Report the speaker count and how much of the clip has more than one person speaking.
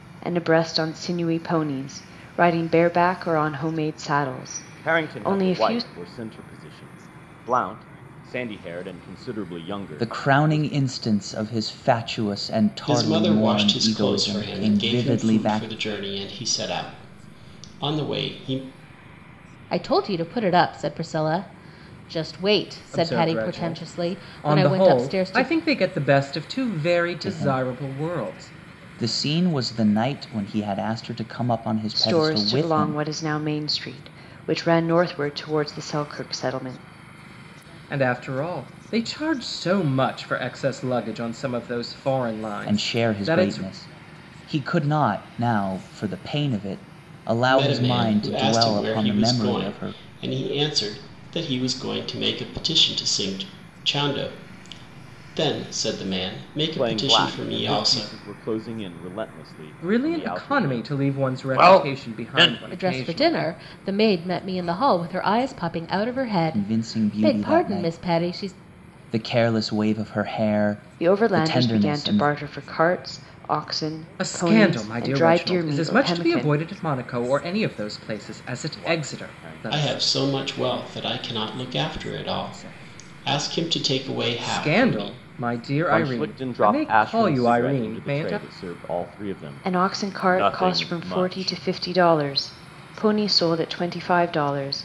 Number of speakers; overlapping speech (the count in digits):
6, about 35%